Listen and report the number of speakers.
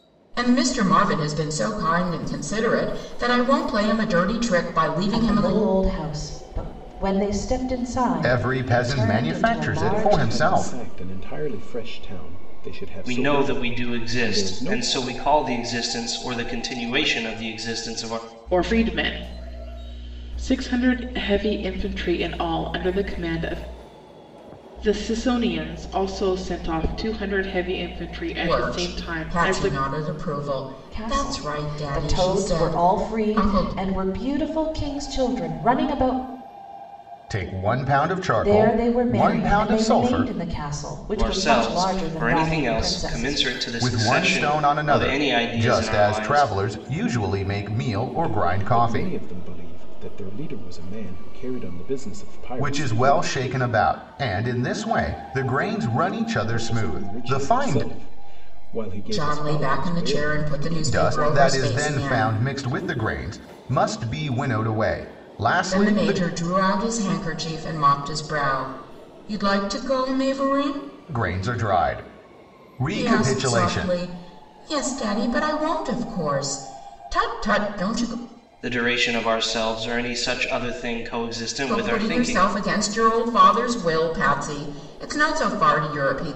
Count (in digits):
6